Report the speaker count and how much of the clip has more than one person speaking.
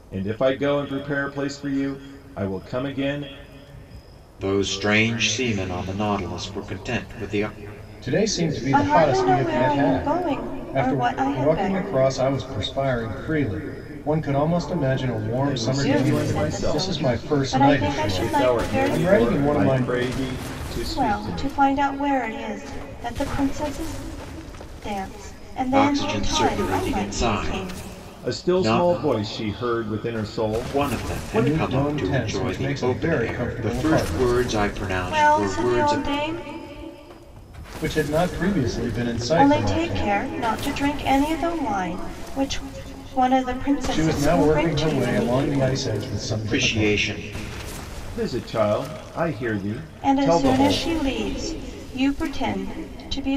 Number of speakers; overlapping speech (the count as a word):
four, about 38%